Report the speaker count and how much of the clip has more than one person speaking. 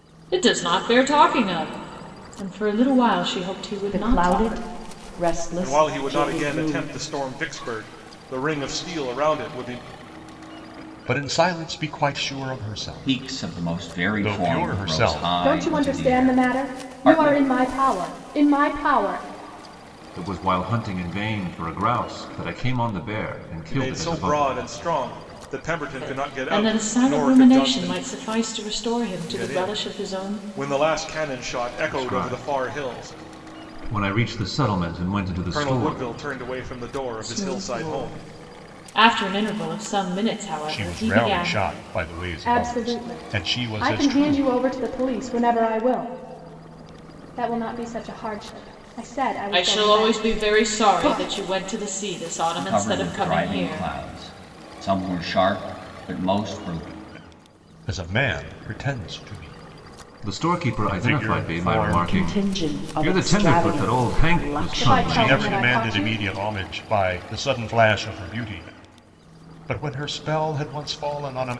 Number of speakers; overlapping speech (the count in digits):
7, about 36%